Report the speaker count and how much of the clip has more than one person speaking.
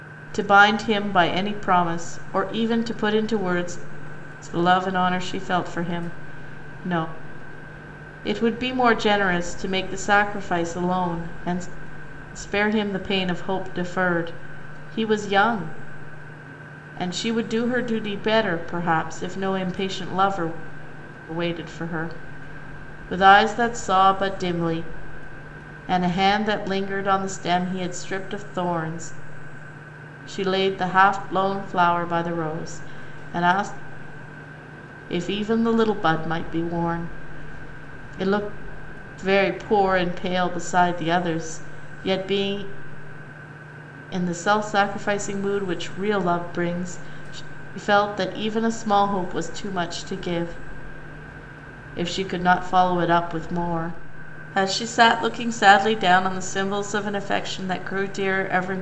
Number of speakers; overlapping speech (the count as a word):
one, no overlap